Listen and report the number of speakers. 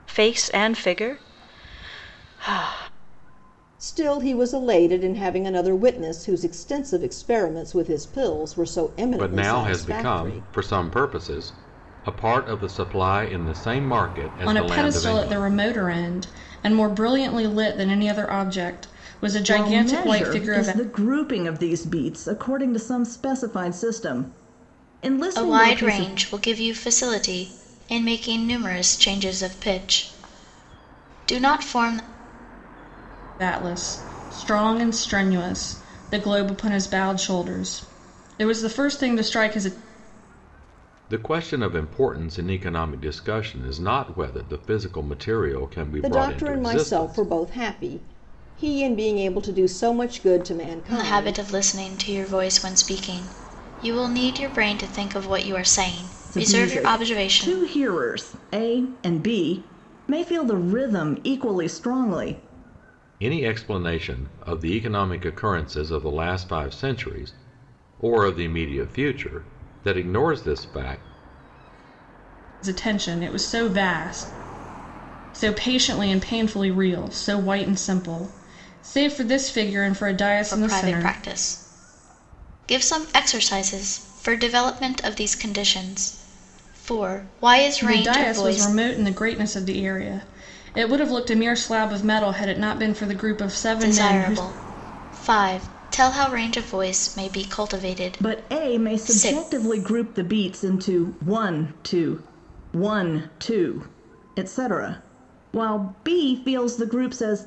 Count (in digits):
6